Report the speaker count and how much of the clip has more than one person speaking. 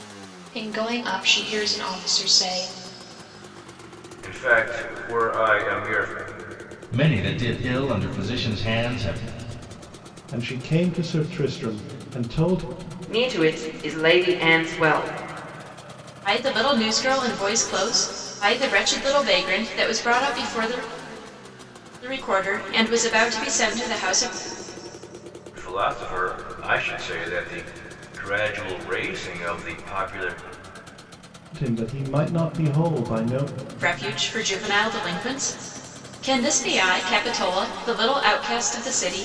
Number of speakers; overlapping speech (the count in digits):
6, no overlap